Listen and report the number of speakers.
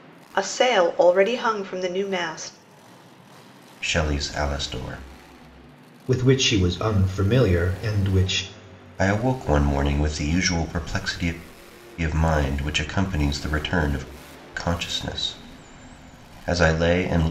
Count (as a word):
three